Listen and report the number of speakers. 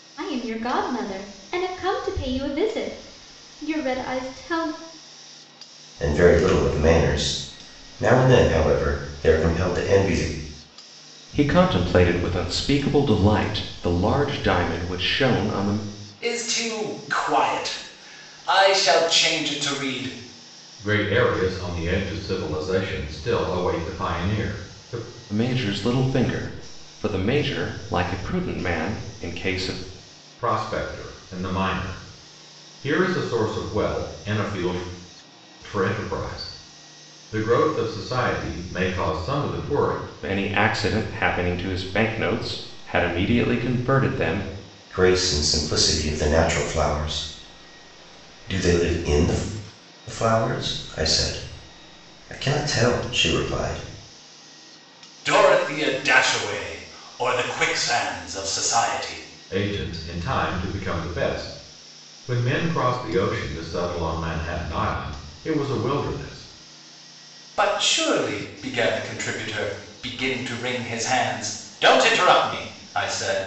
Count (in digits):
5